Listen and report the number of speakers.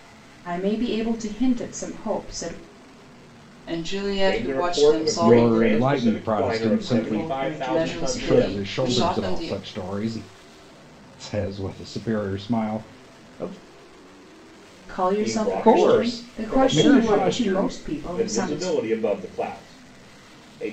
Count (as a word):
four